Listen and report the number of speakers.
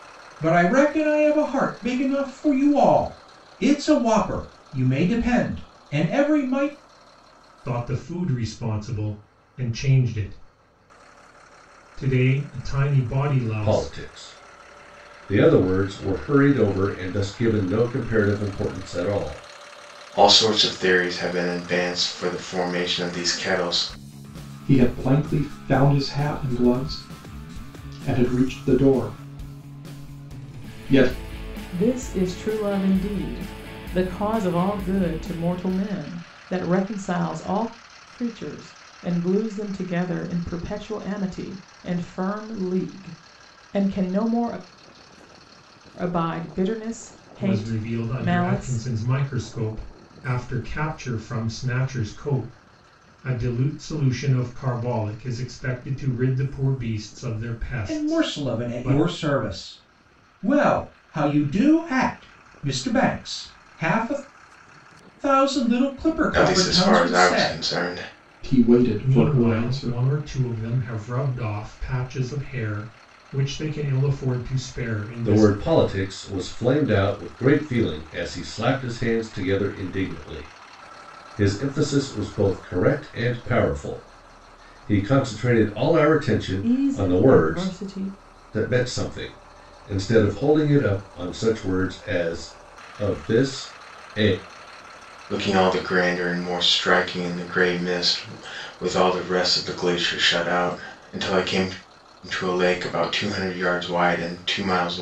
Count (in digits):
6